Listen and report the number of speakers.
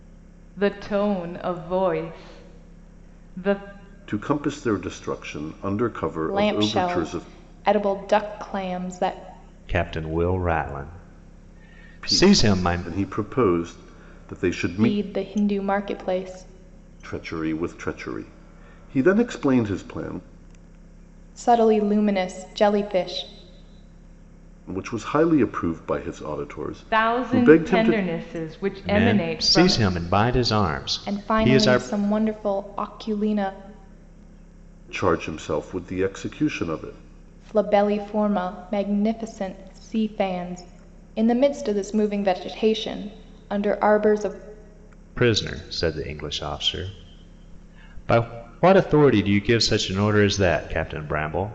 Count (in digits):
4